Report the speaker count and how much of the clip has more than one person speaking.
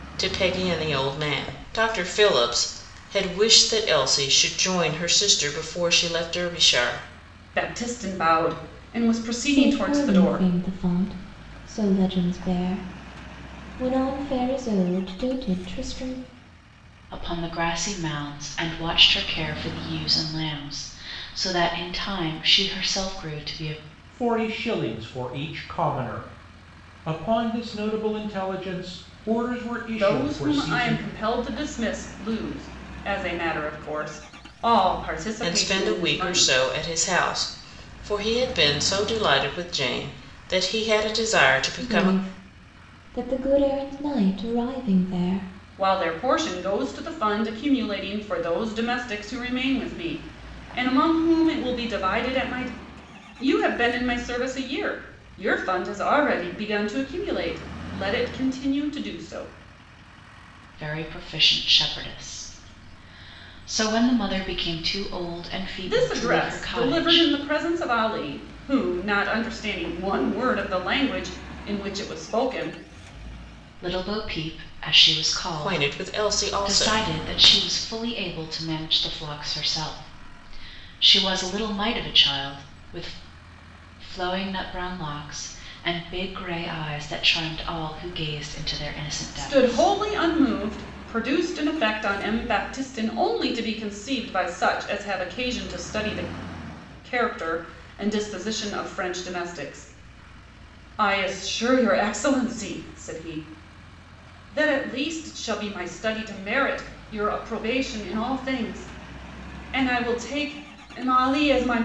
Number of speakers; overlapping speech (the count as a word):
five, about 6%